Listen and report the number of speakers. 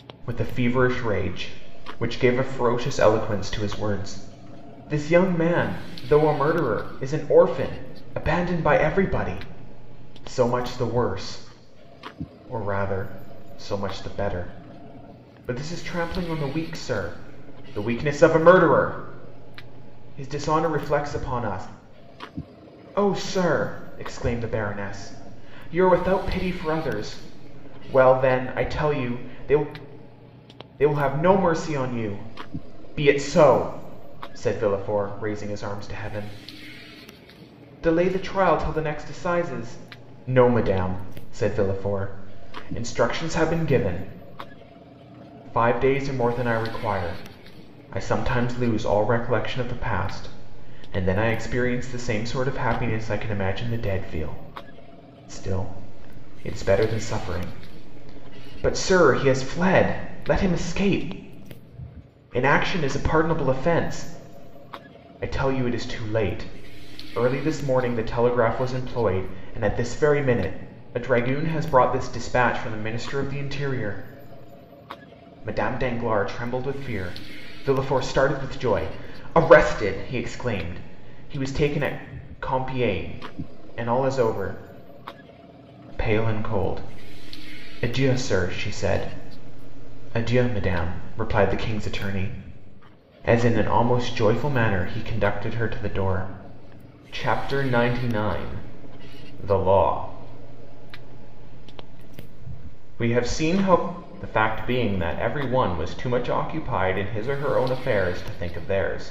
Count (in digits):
1